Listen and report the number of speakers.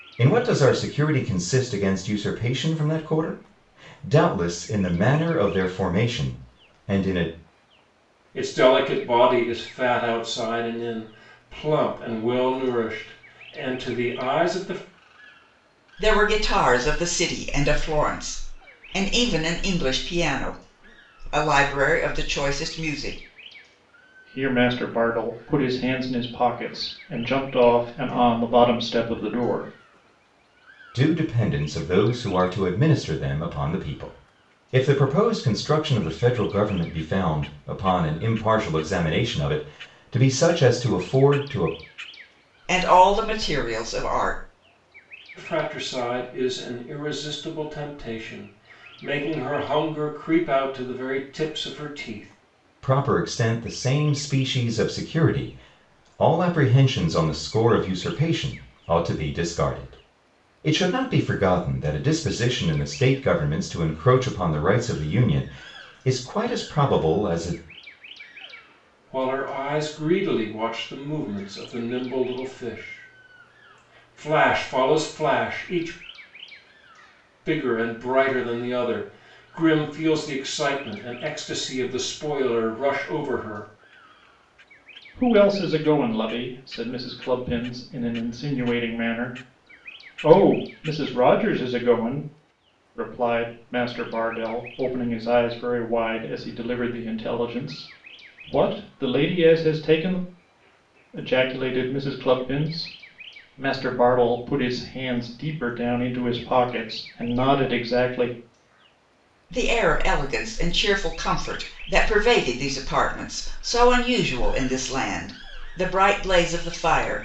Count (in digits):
4